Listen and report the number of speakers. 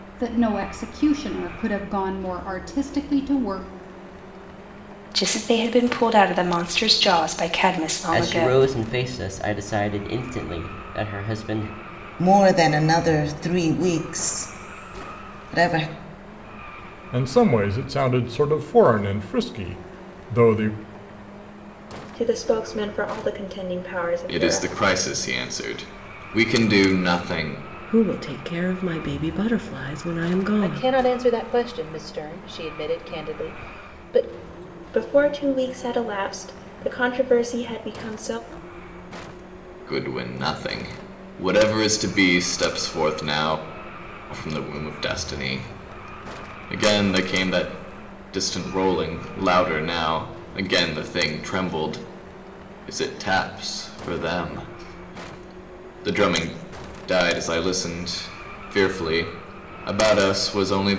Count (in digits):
9